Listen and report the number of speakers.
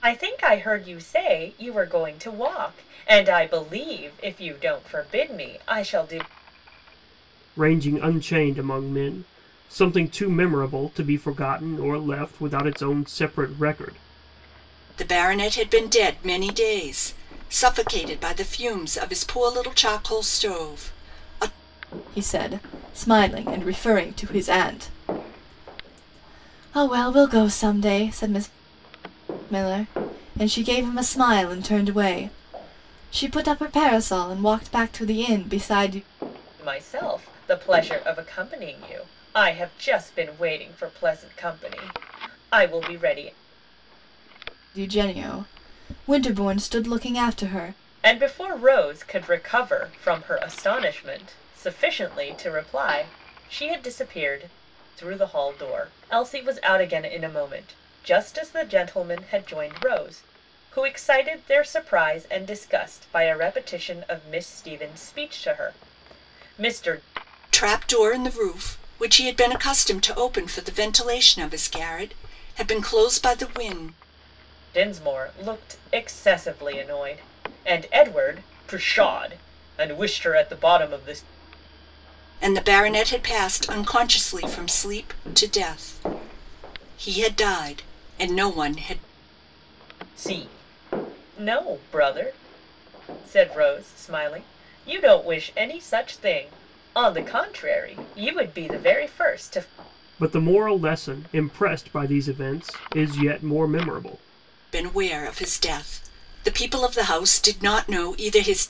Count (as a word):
four